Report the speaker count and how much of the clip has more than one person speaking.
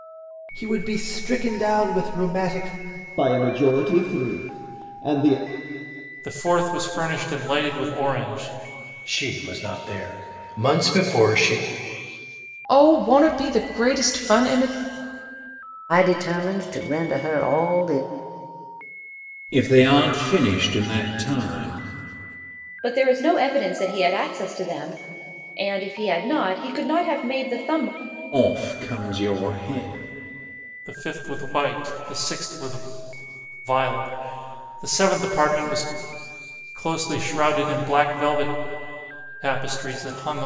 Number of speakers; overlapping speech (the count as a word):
eight, no overlap